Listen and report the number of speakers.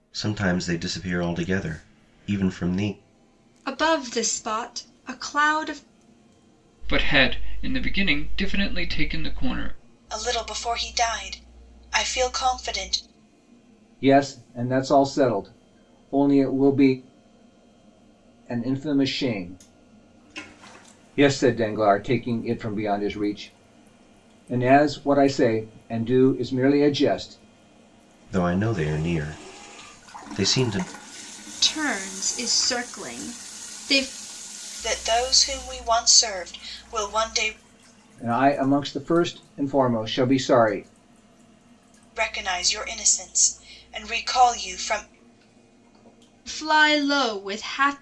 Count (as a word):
five